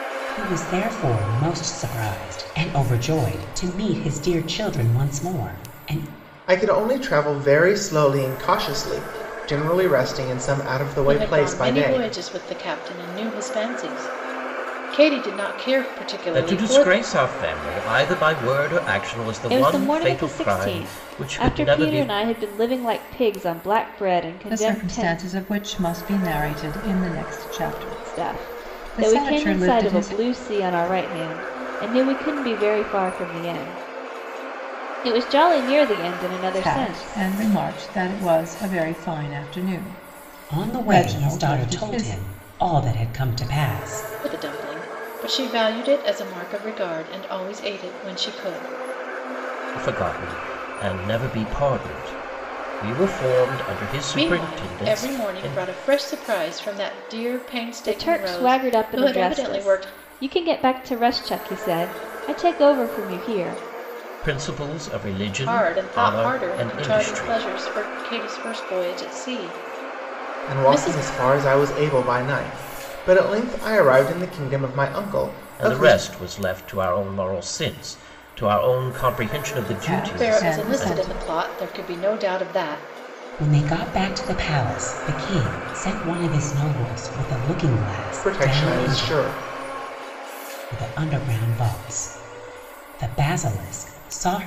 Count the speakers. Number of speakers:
6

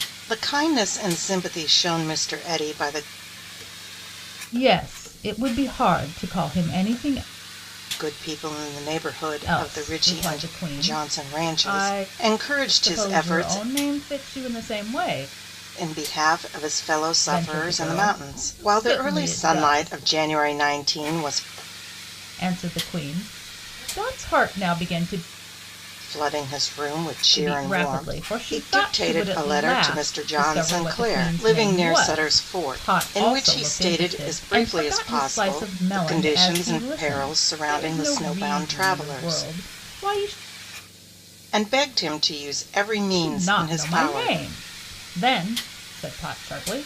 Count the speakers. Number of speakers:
2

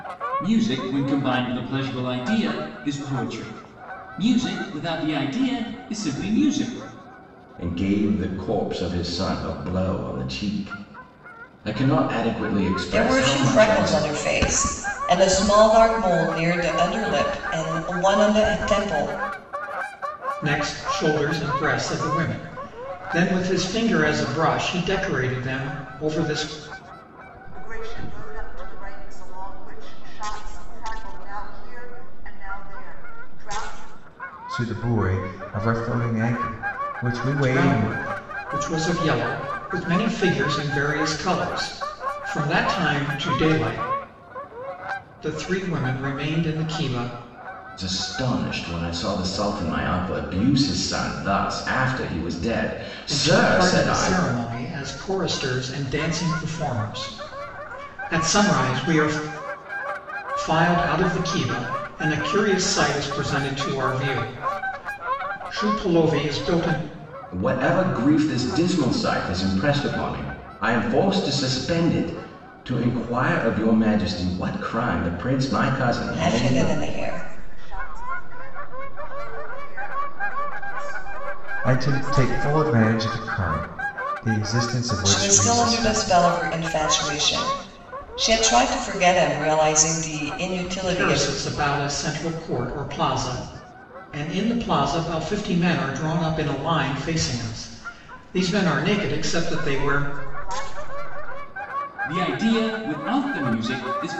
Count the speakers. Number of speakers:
6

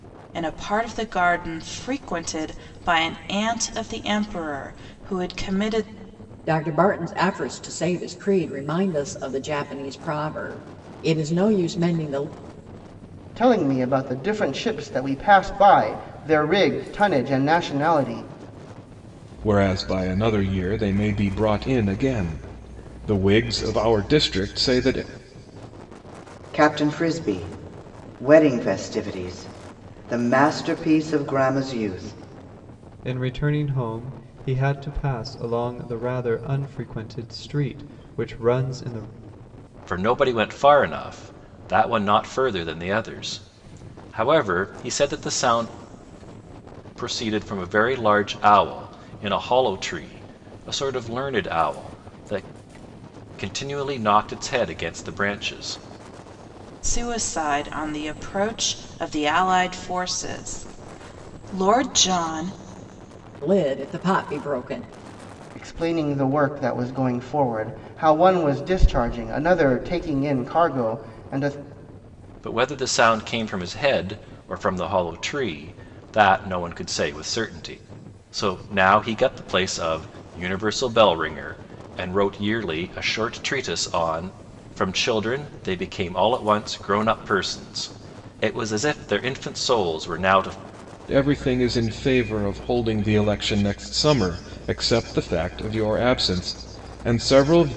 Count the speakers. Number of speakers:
7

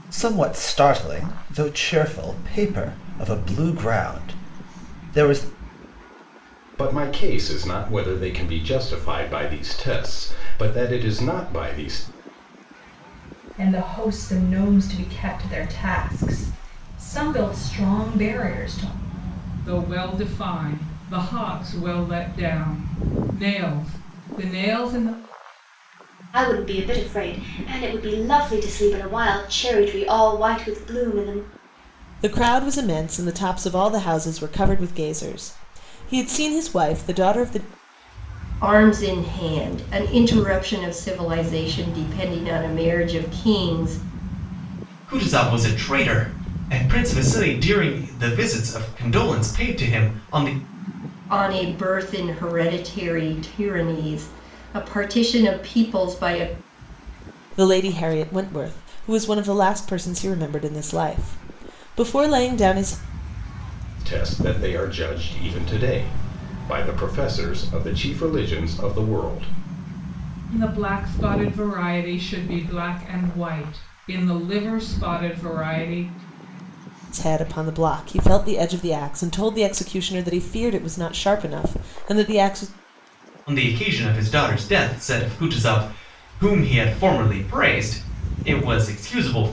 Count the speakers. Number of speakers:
8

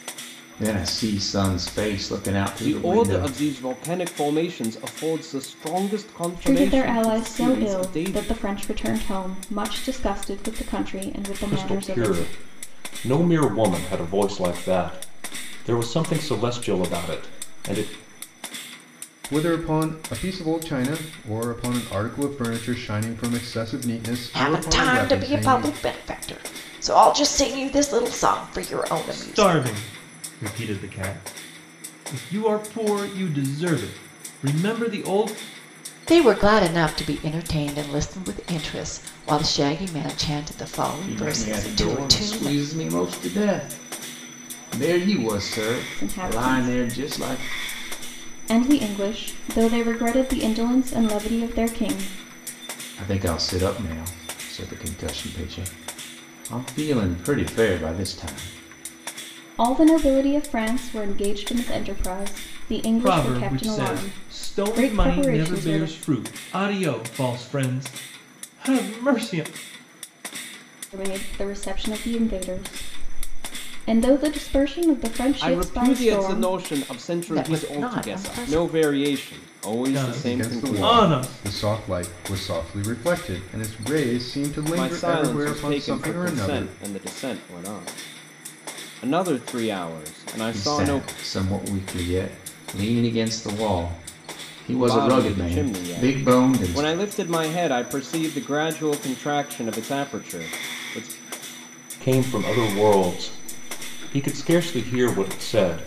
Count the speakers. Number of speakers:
7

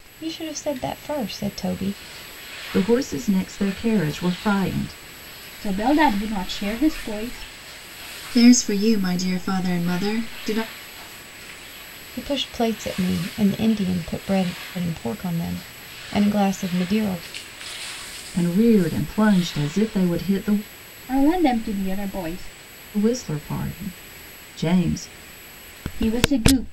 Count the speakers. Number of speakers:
4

